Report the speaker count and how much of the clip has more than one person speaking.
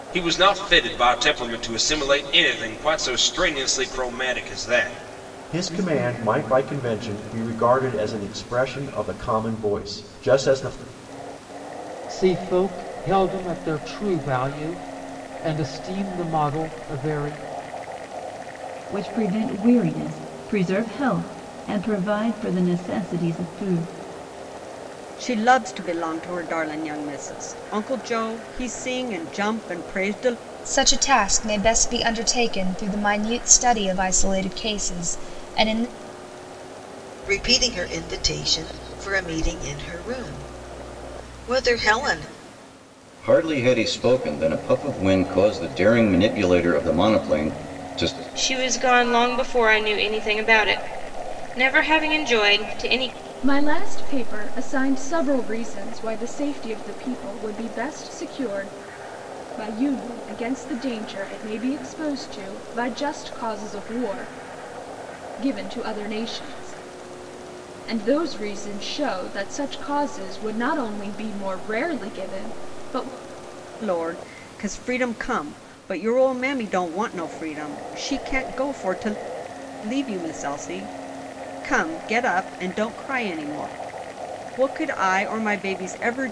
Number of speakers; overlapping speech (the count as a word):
ten, no overlap